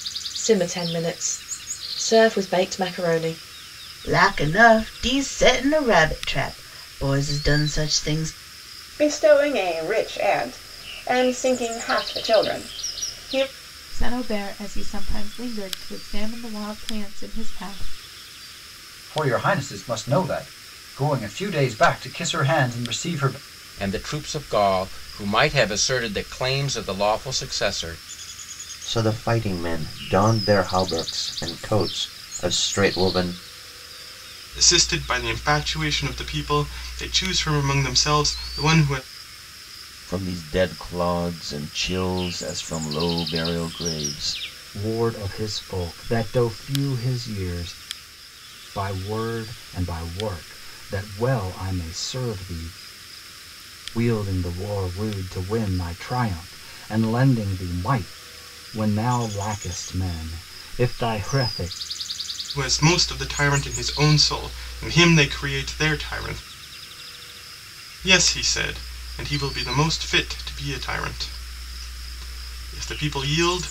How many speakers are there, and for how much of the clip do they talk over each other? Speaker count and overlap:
10, no overlap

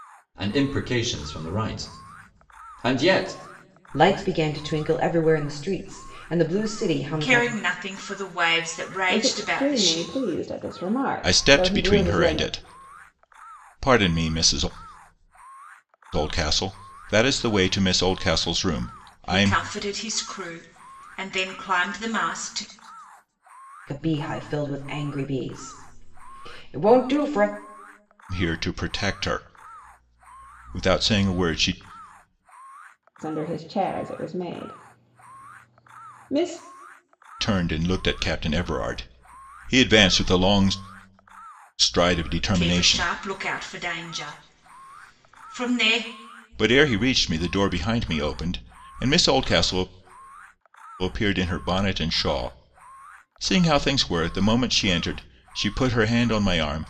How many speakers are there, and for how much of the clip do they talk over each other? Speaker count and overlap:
5, about 7%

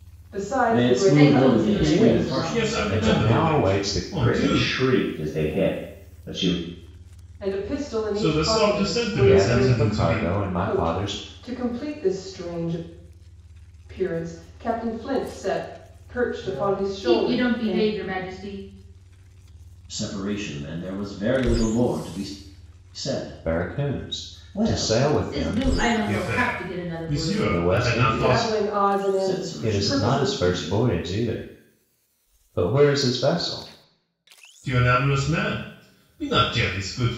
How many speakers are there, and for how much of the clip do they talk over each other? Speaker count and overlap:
6, about 41%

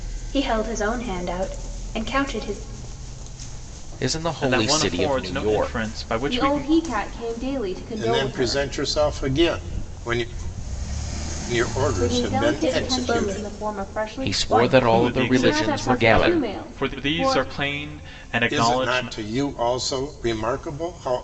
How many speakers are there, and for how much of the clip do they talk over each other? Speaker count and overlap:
5, about 42%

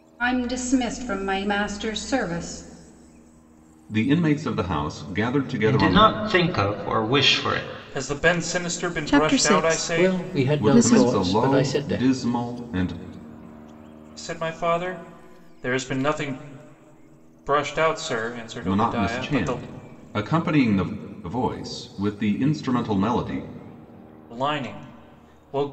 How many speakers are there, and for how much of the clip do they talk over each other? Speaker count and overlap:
6, about 18%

